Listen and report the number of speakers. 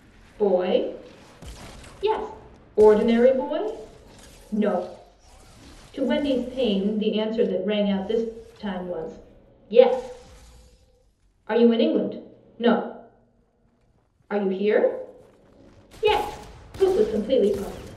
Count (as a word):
one